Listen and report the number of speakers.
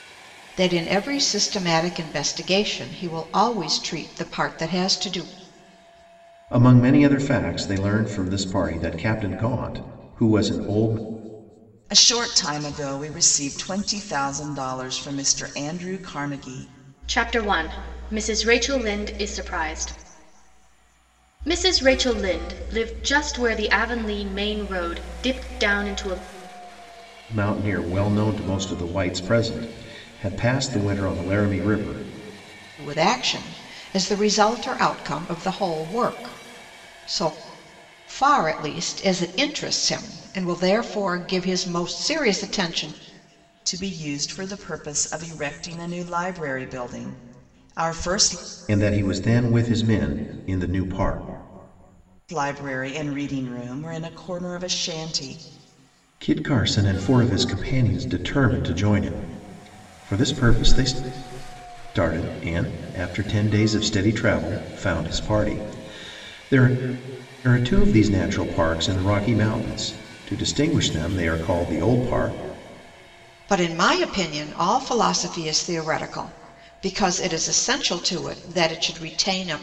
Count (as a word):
four